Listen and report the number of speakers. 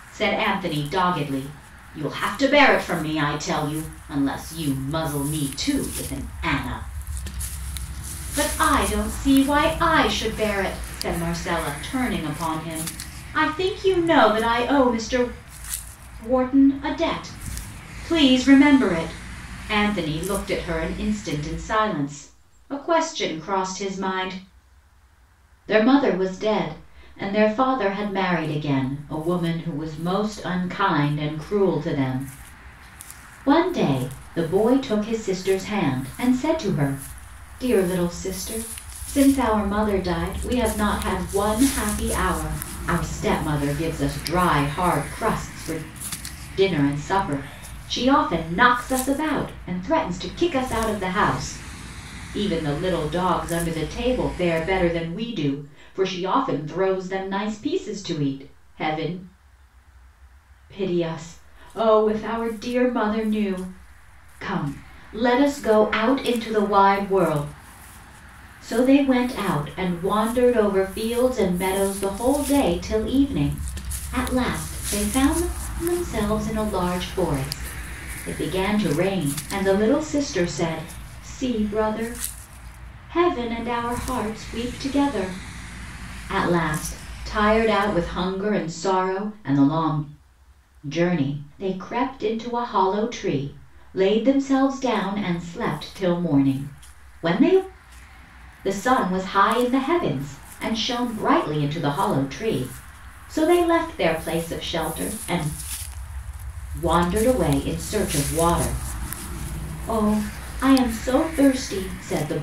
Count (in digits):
1